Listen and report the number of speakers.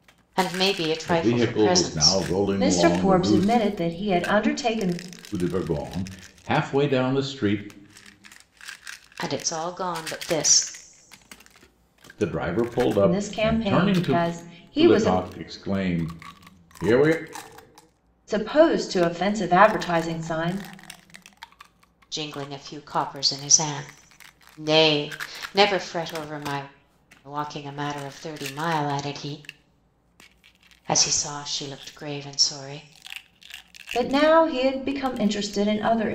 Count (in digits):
3